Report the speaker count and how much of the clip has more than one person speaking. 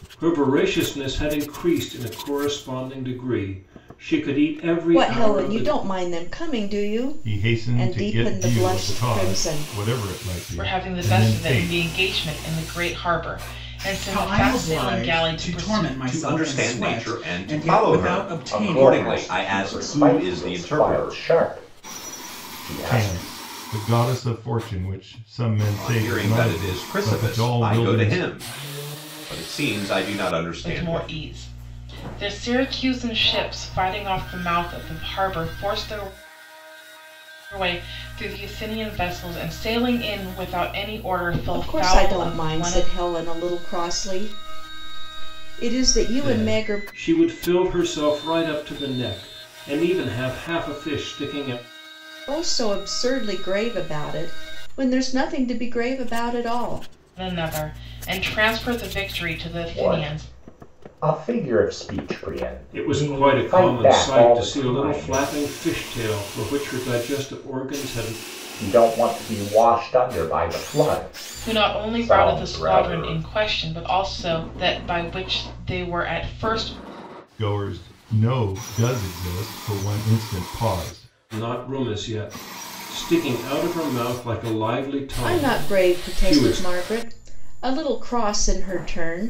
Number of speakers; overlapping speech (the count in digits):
7, about 27%